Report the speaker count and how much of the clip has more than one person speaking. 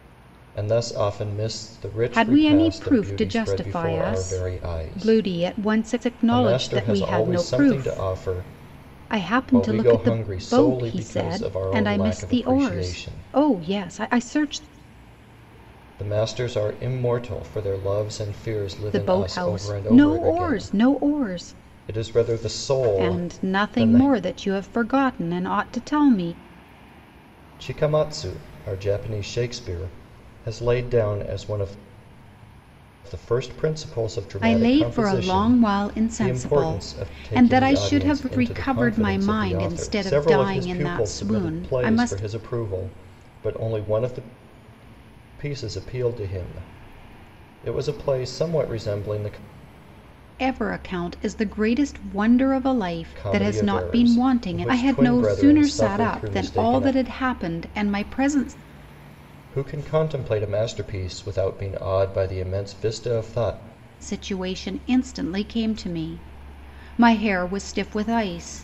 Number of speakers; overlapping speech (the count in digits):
2, about 37%